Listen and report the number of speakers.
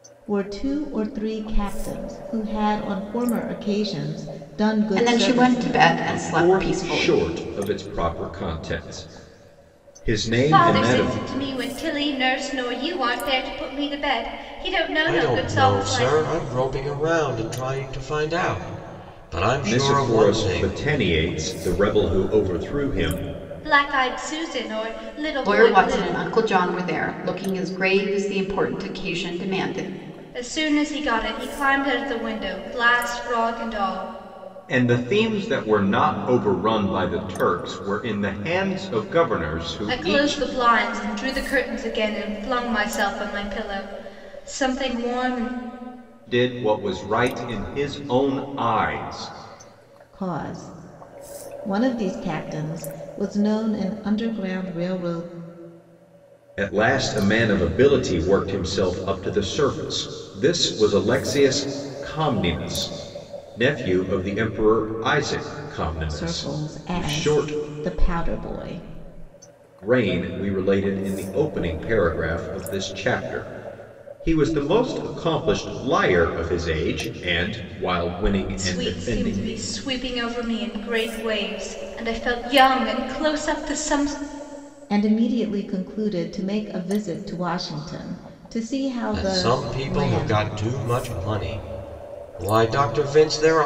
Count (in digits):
5